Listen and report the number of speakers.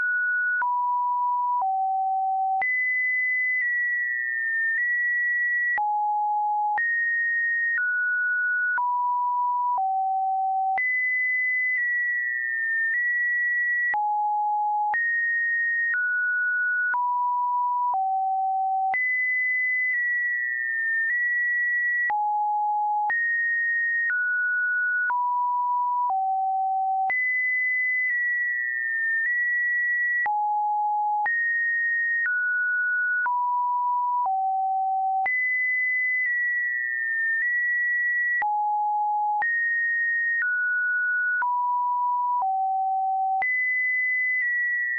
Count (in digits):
0